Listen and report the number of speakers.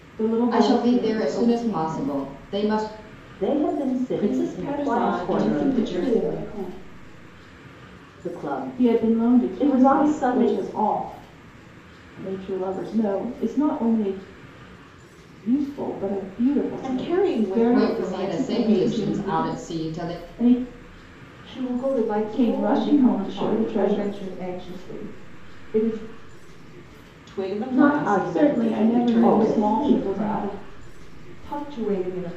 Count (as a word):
six